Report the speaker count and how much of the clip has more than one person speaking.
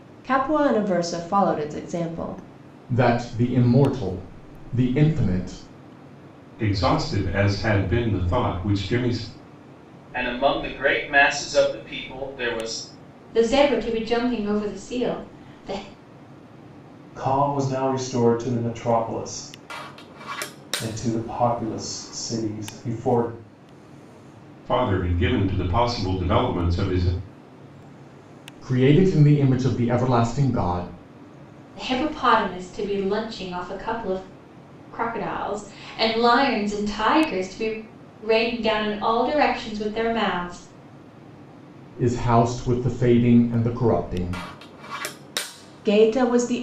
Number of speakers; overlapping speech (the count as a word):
six, no overlap